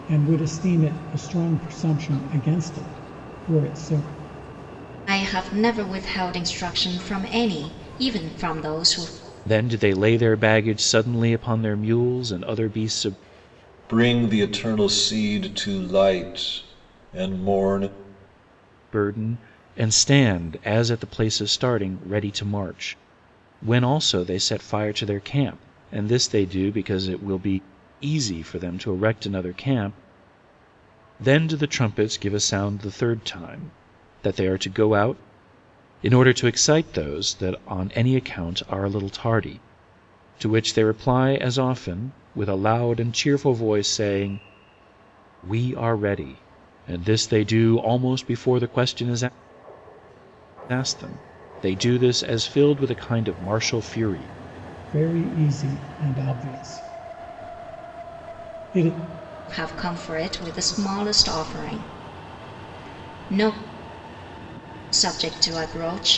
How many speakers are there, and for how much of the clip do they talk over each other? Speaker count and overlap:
four, no overlap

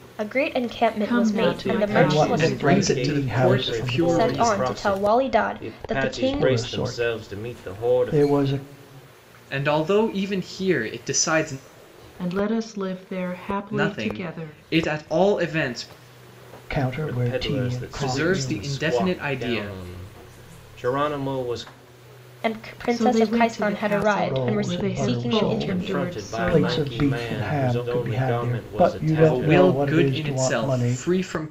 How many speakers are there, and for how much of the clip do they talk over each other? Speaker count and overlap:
five, about 60%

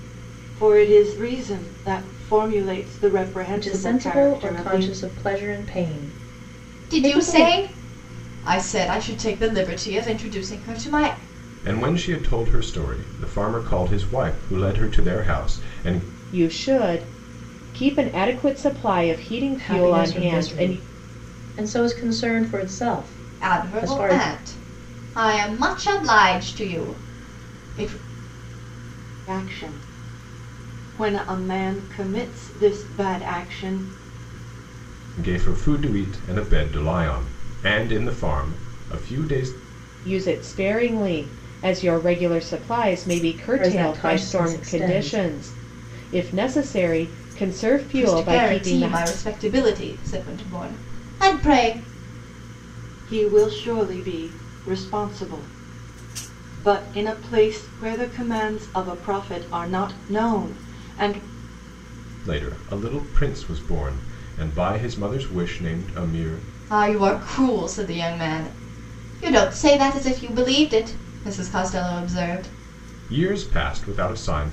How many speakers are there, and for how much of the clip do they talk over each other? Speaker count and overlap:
five, about 9%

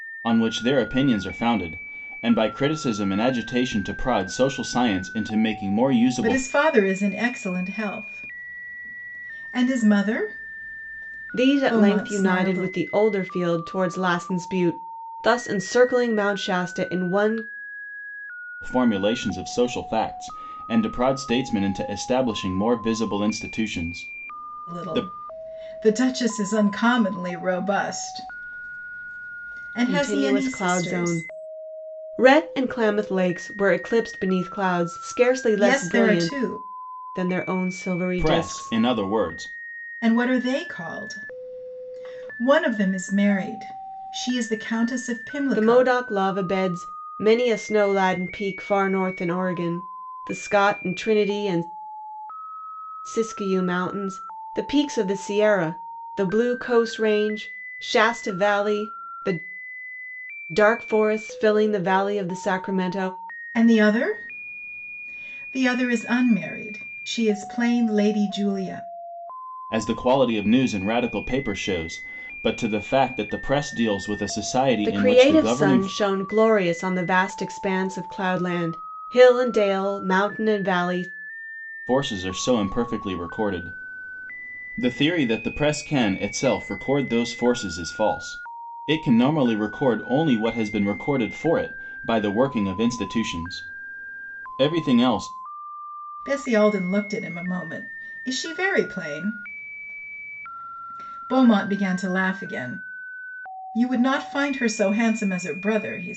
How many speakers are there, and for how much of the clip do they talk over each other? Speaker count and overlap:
three, about 6%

